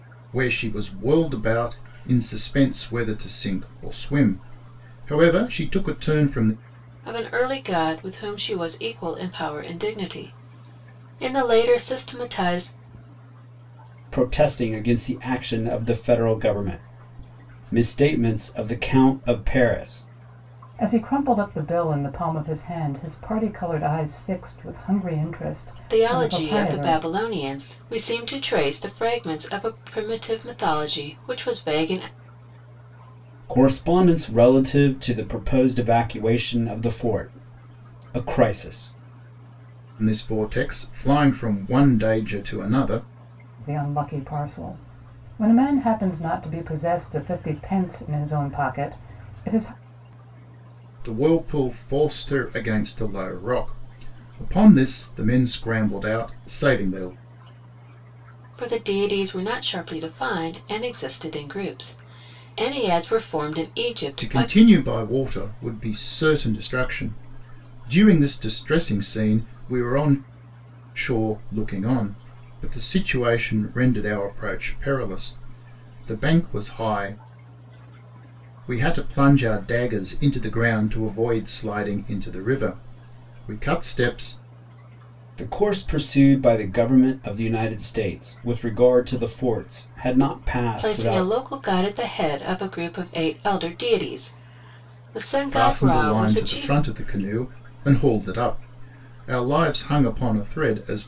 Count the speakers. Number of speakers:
4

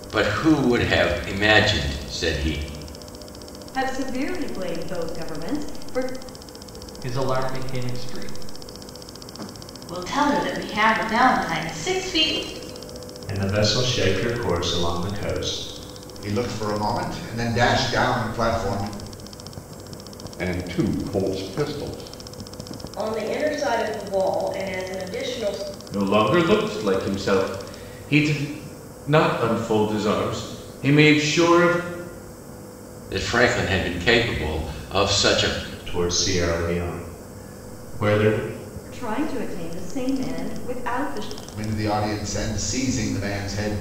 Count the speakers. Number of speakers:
9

